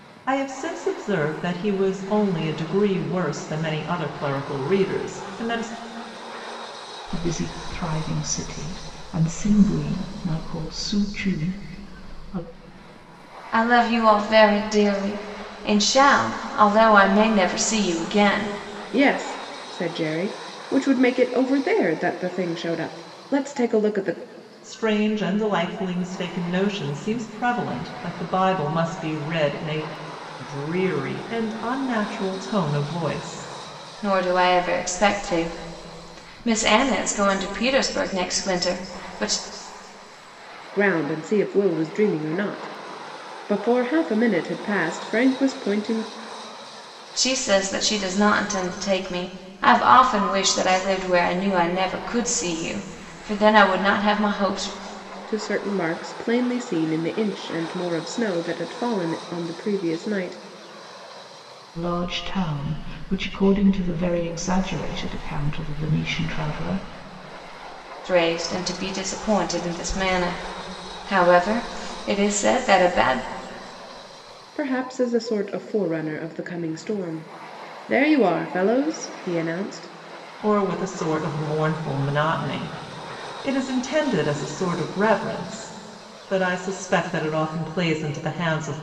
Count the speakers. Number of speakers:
4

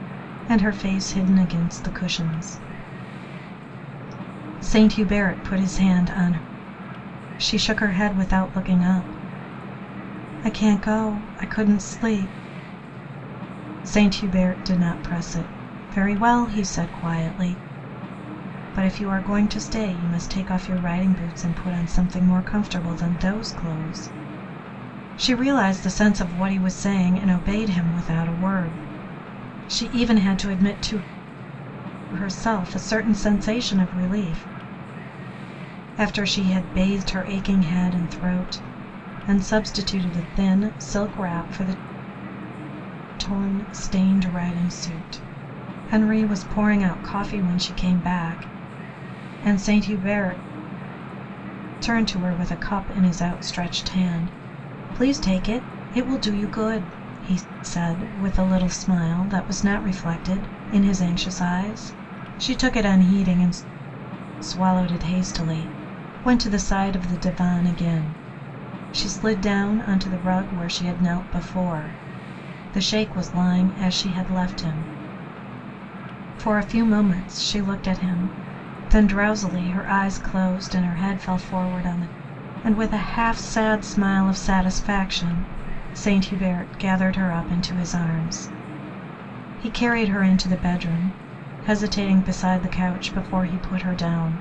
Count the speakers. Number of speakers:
1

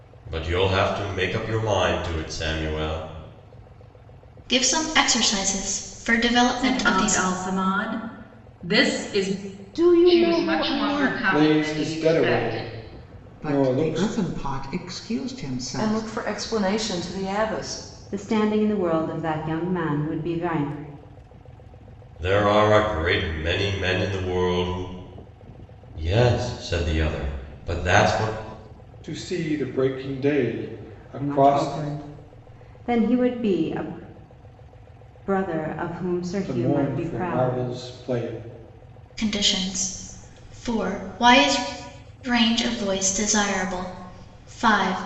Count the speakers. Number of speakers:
9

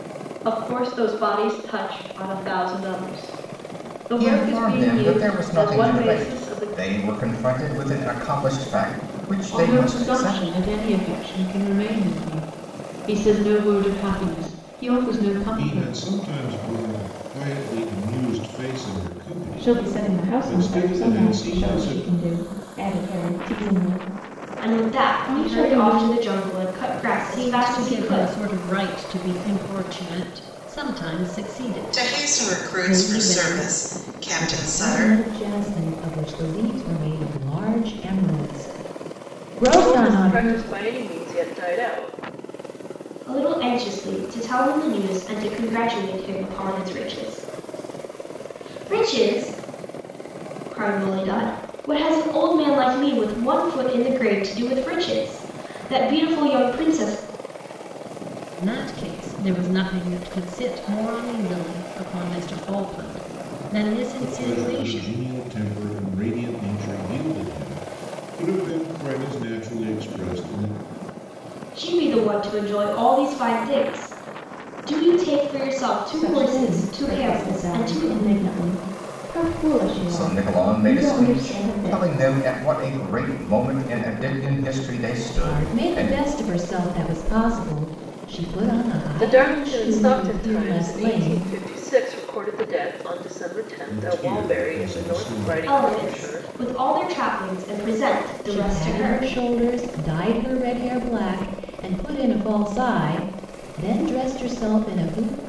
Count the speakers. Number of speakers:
10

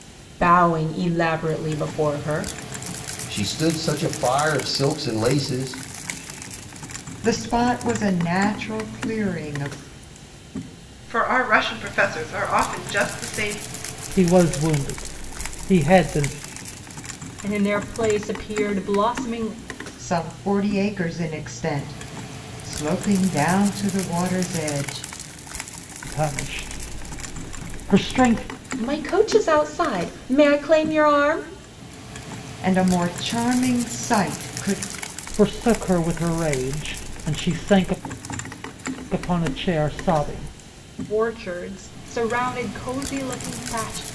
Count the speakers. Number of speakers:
6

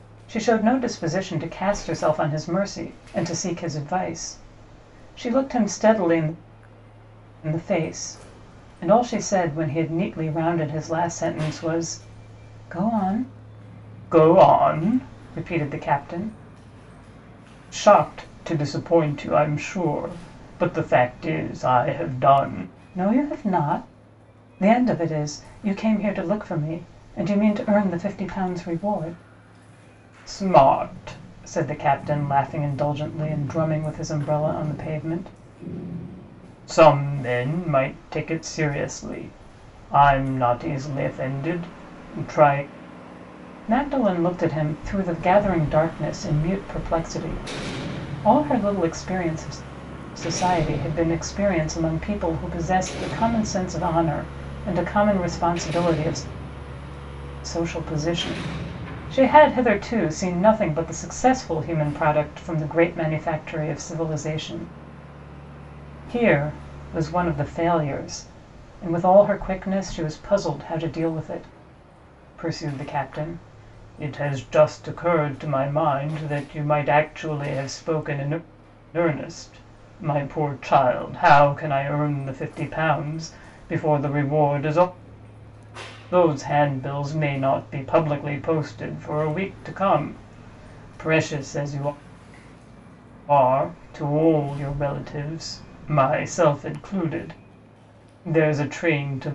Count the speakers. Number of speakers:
1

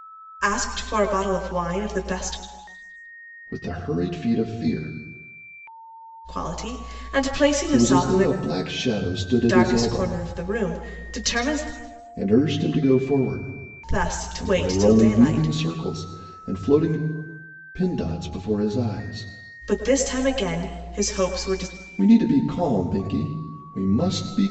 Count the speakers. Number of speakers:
2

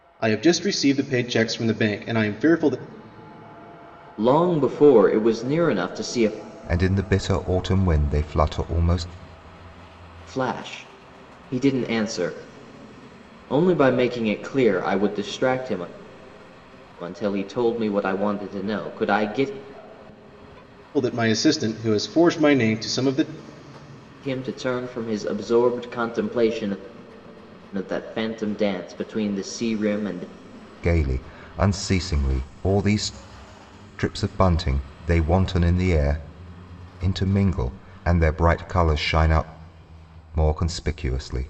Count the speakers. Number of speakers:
3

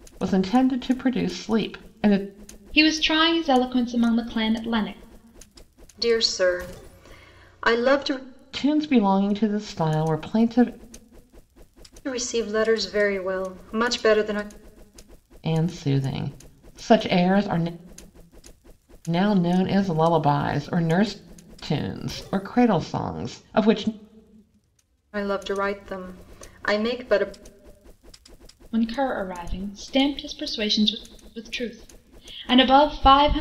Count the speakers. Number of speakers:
3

